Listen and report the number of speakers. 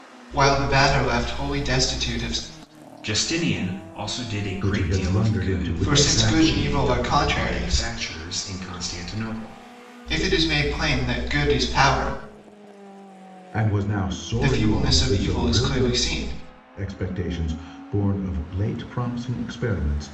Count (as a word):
three